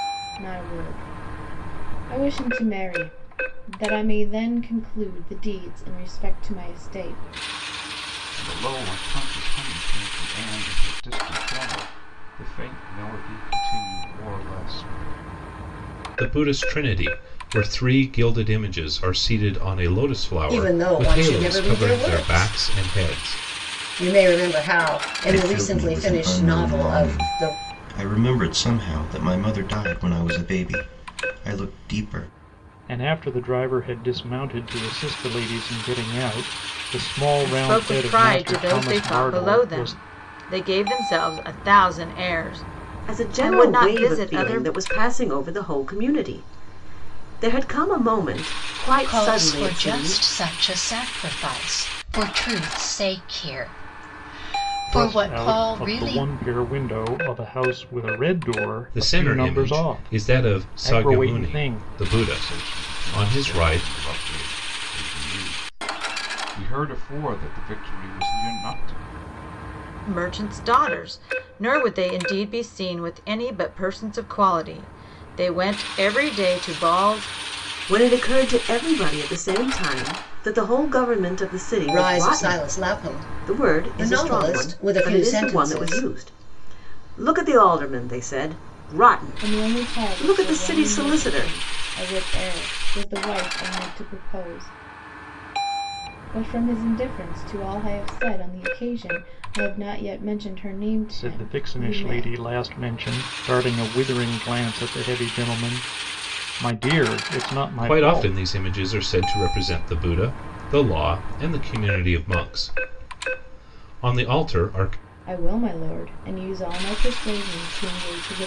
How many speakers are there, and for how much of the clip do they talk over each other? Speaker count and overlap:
nine, about 21%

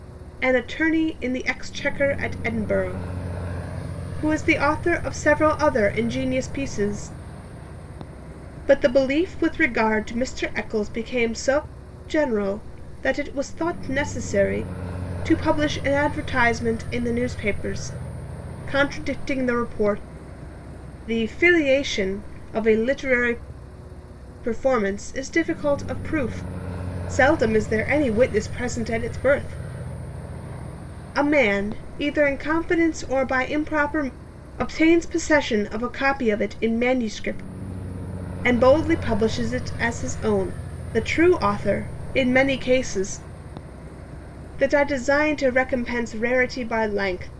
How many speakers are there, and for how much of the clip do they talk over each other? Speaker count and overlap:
one, no overlap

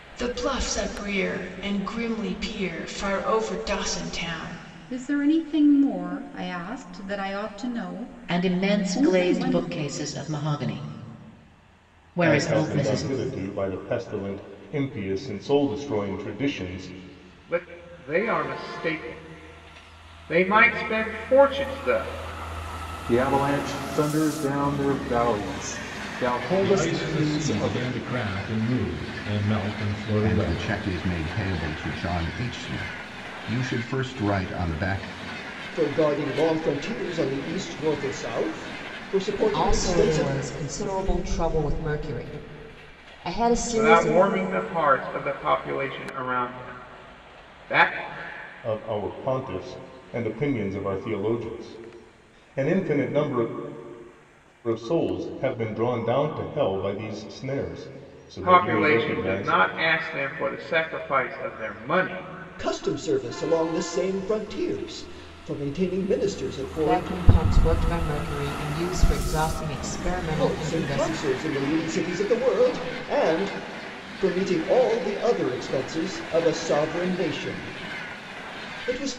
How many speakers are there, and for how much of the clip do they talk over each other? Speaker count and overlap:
ten, about 10%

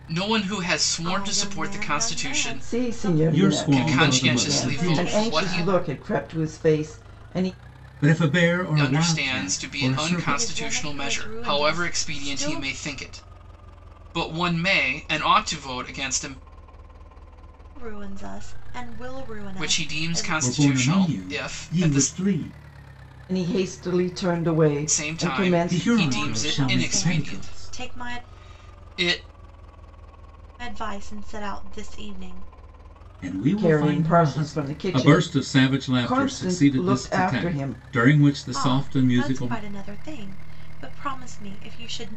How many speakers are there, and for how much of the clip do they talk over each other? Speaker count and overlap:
four, about 46%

